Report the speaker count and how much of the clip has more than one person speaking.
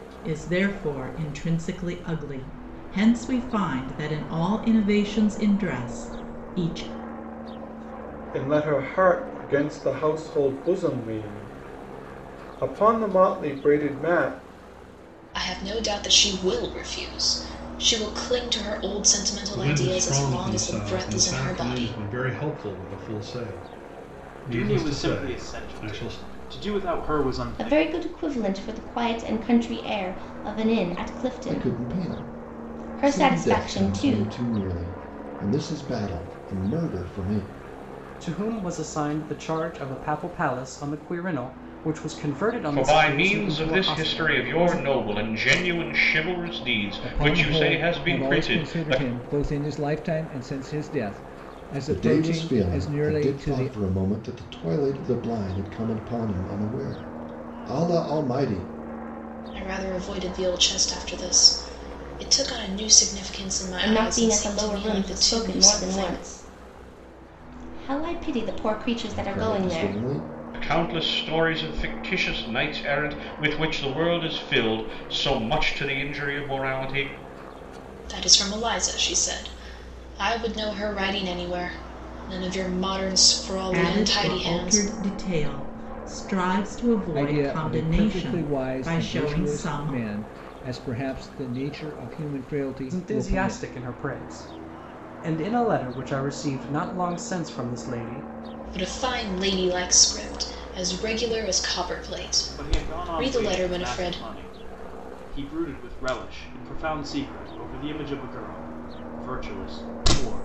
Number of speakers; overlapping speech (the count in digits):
10, about 22%